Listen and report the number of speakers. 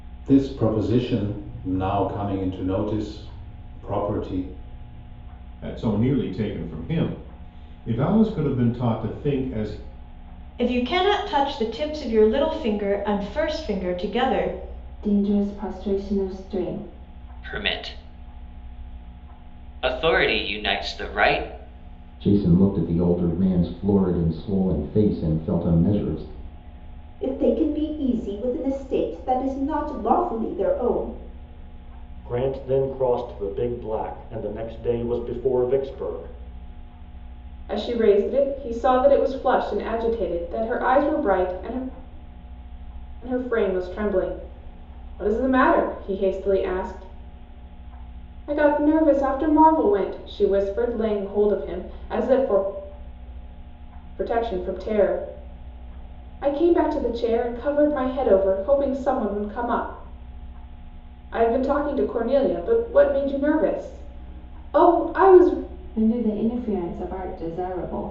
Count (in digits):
9